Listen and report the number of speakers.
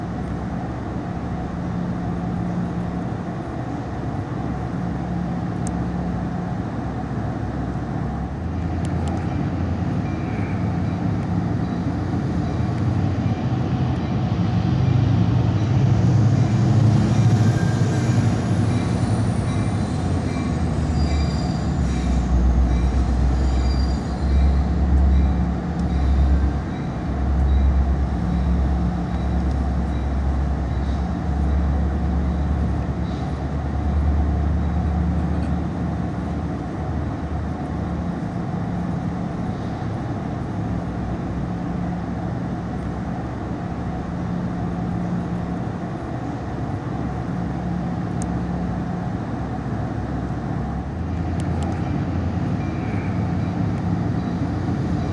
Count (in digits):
0